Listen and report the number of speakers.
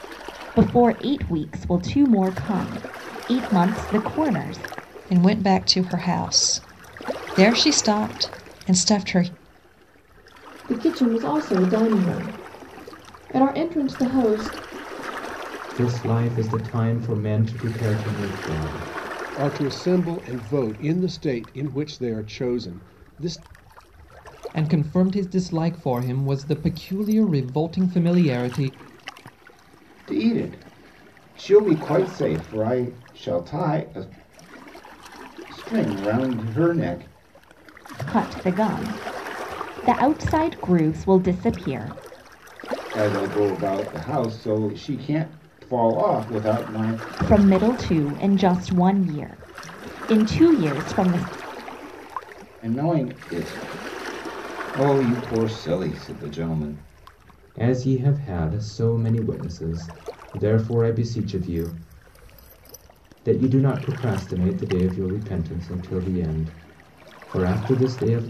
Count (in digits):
7